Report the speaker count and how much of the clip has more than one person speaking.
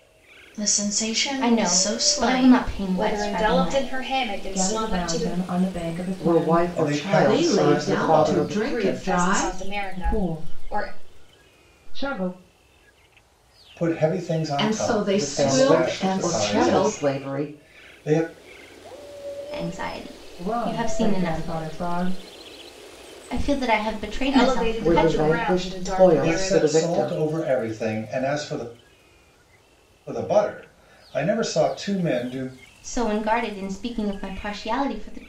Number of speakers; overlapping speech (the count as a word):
seven, about 41%